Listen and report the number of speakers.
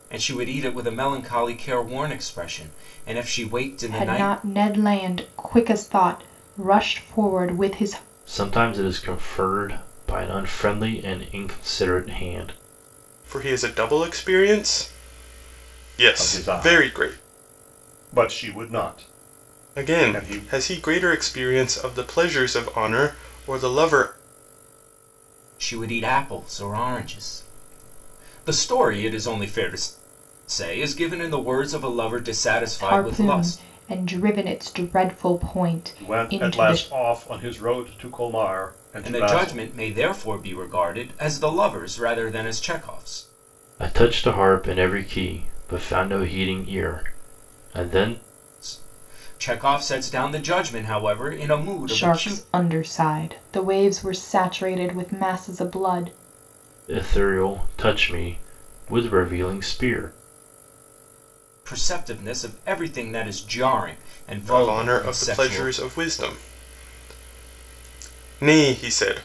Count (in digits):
5